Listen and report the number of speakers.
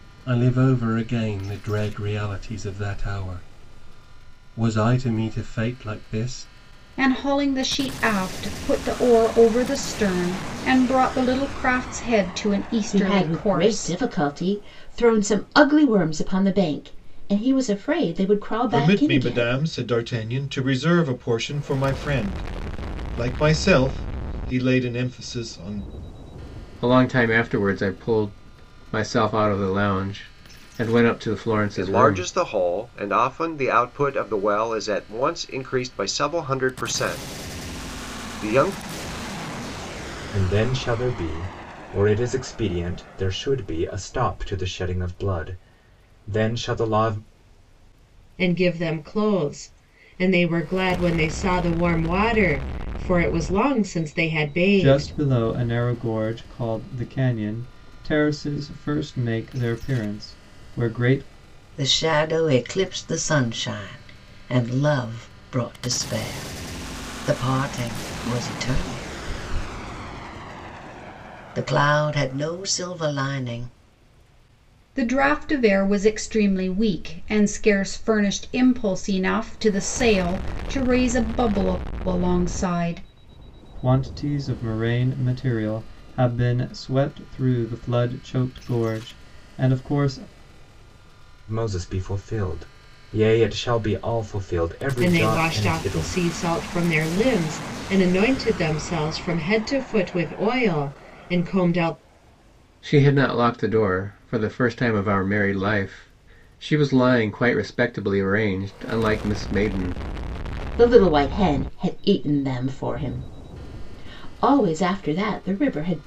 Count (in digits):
10